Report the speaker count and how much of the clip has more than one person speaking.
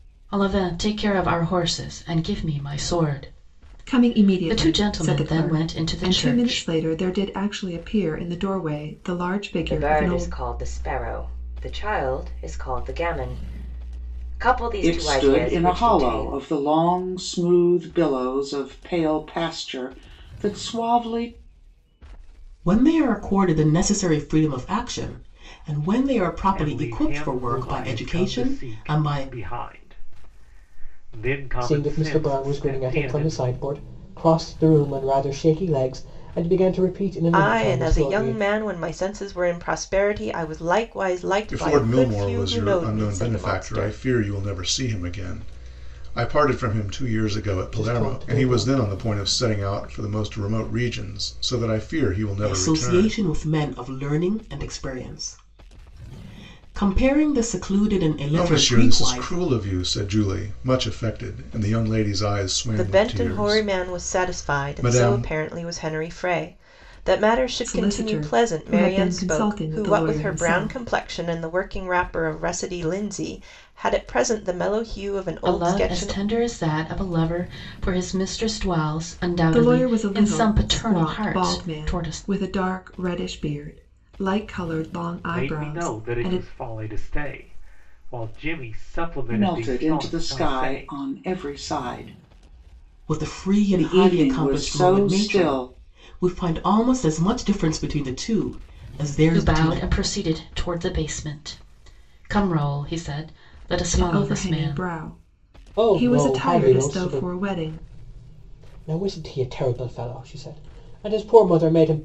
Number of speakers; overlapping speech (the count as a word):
nine, about 31%